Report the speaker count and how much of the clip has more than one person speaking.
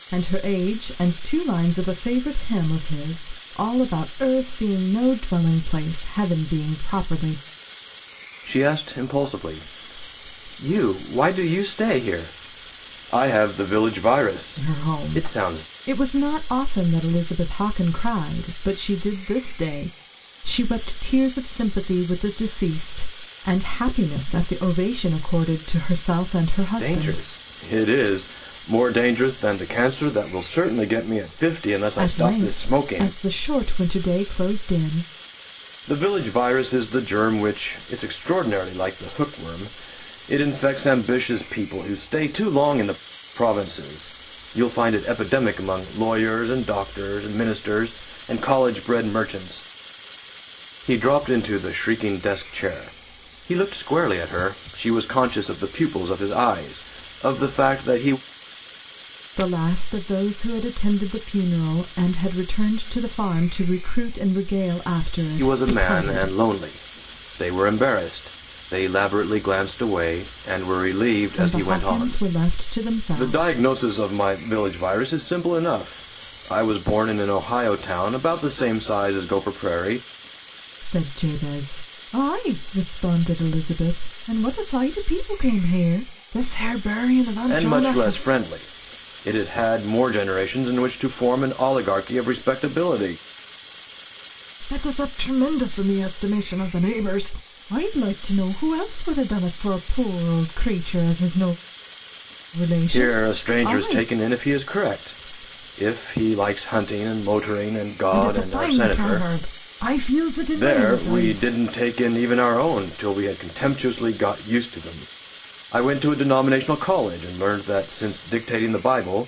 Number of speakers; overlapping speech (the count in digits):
2, about 8%